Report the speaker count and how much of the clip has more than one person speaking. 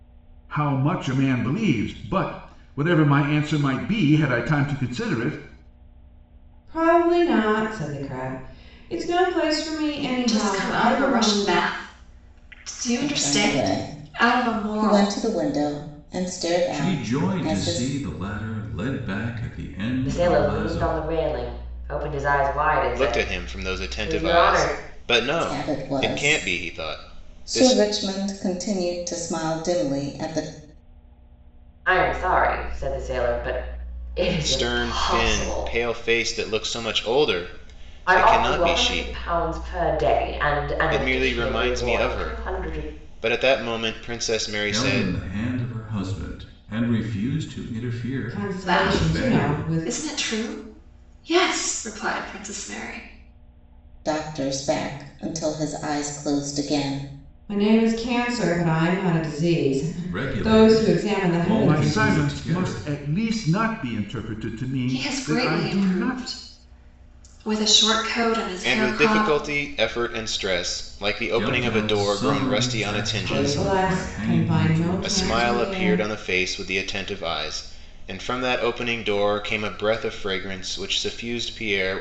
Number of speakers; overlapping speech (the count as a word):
seven, about 32%